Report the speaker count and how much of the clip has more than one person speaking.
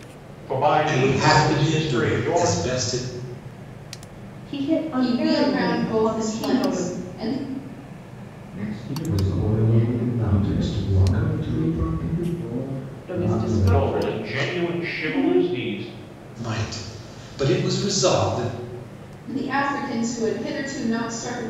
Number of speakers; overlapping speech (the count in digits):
6, about 47%